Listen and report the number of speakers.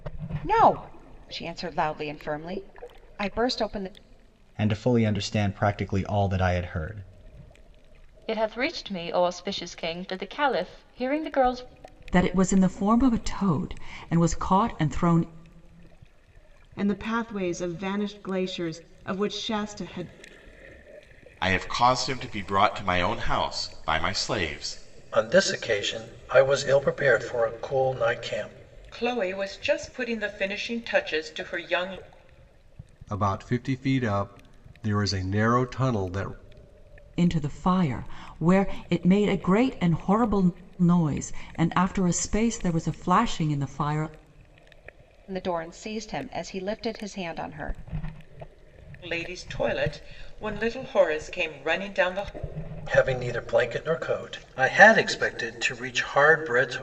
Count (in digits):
9